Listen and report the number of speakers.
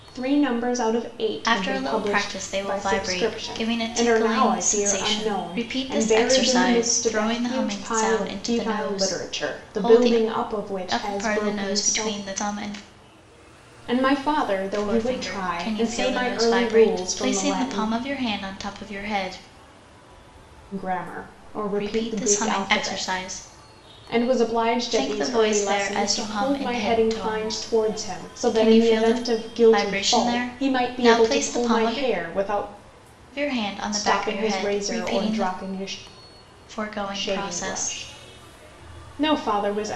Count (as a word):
two